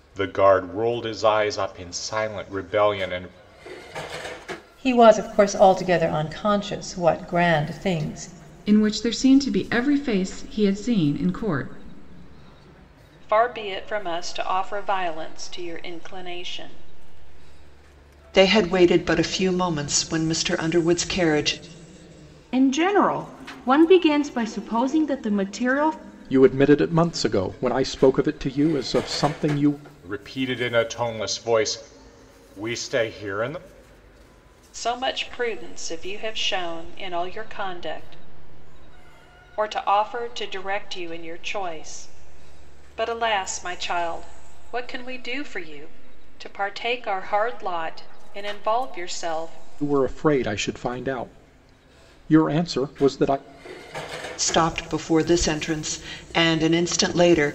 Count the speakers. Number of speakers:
7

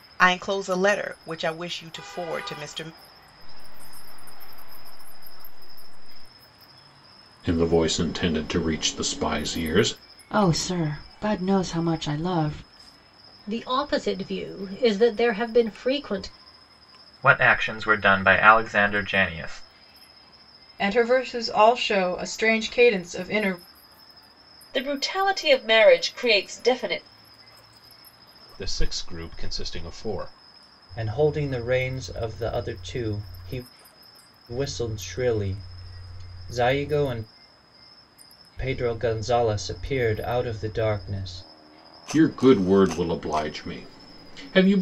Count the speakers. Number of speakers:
10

